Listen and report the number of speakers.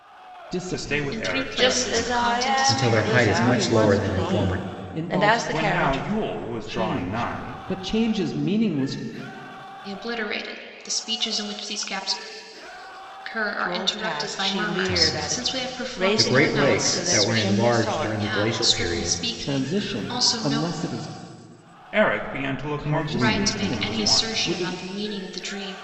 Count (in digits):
5